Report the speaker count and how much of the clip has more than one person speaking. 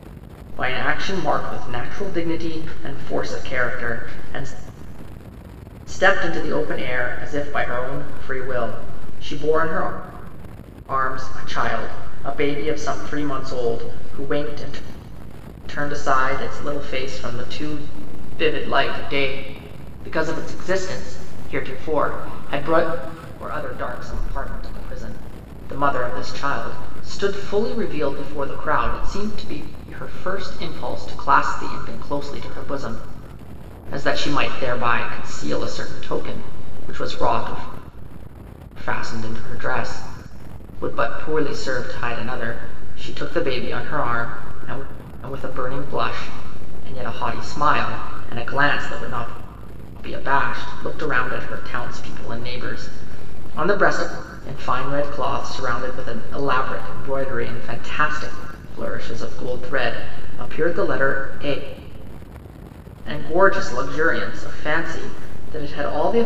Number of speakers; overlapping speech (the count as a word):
one, no overlap